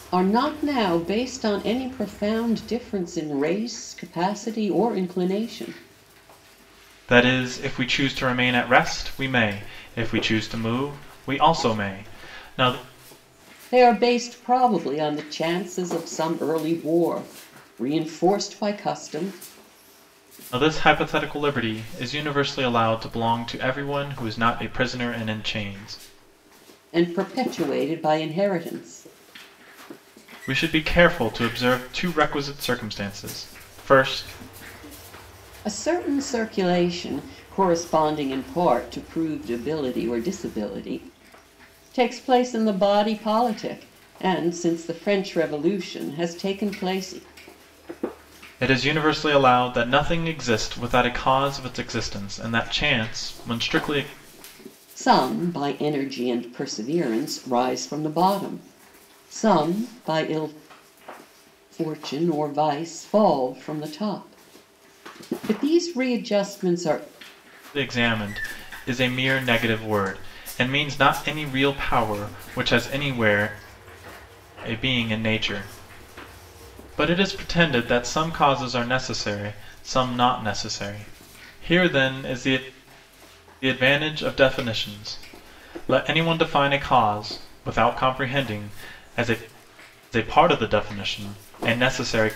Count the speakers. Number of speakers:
2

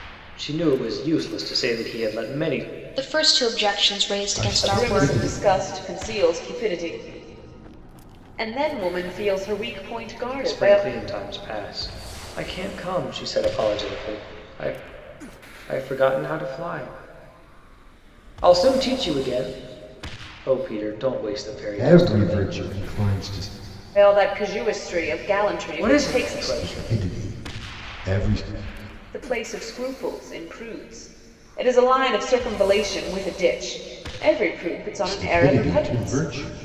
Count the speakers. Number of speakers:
4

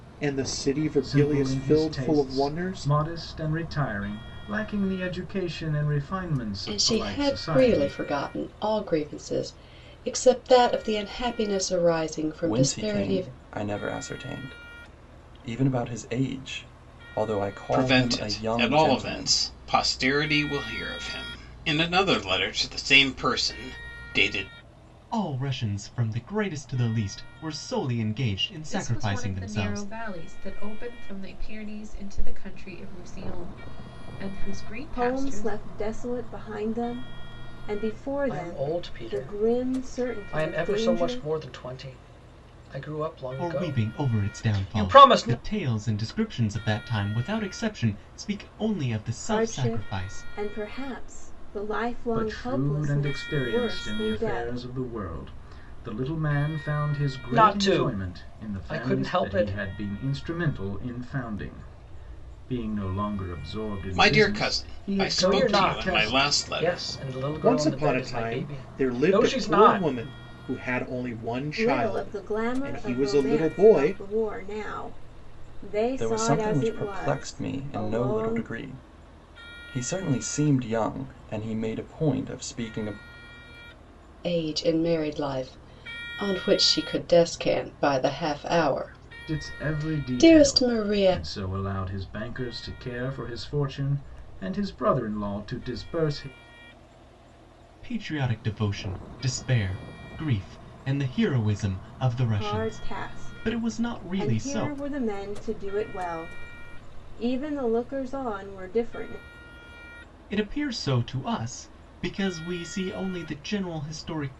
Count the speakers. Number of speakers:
9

